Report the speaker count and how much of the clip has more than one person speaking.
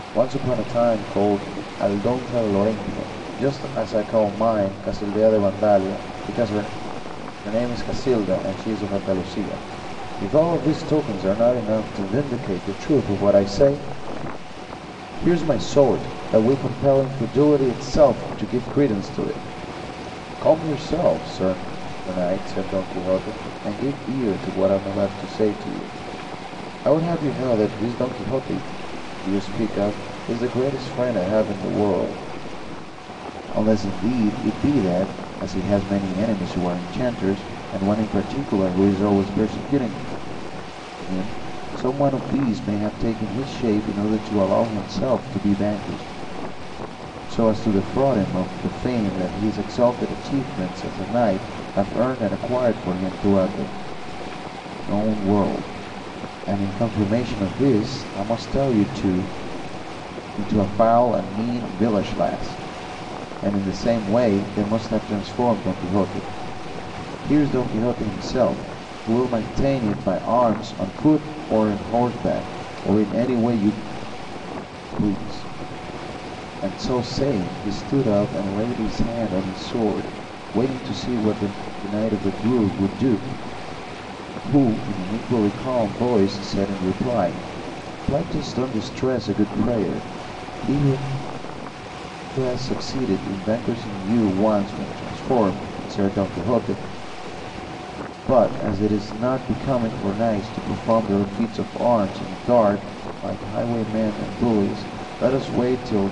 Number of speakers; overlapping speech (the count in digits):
1, no overlap